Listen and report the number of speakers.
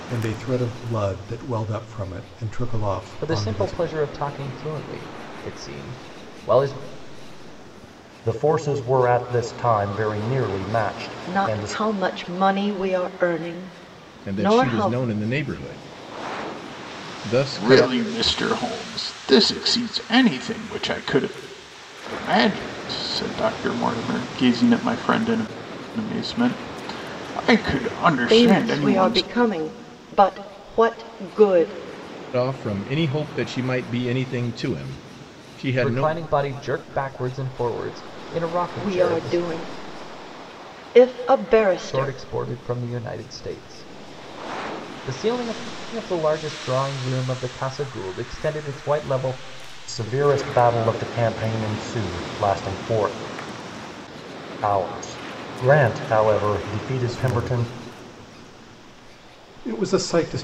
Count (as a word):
six